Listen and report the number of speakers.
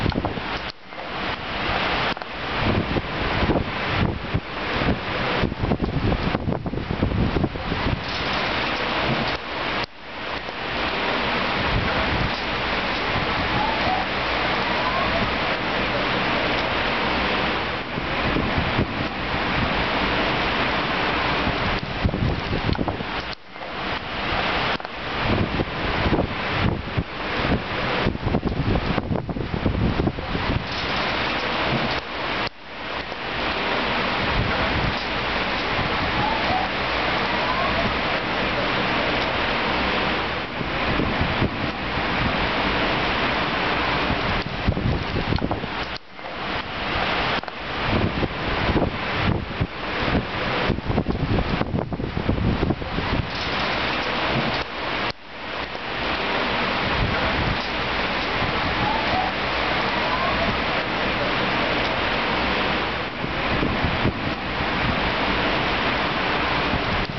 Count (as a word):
zero